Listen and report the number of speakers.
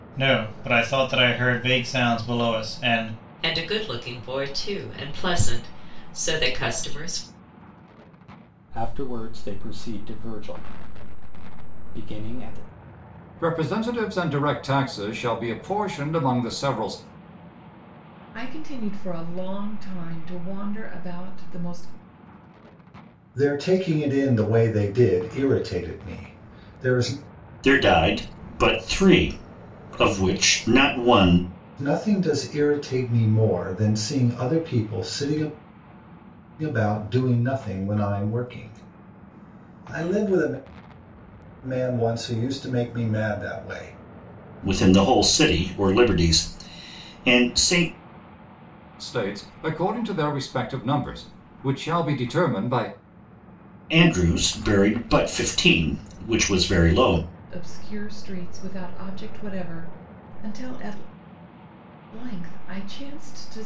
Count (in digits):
7